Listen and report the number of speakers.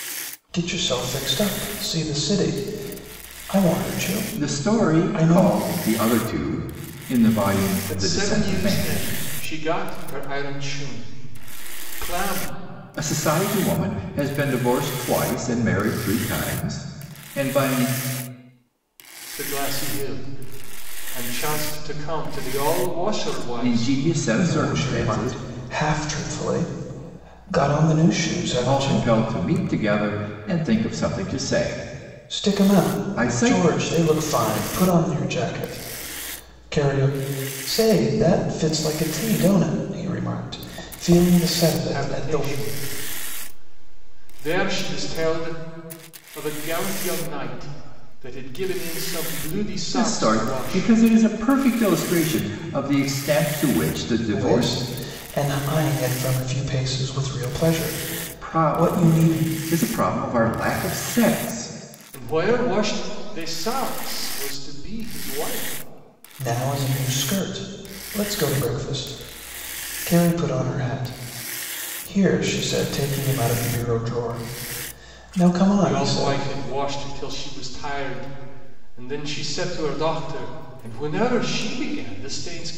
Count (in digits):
3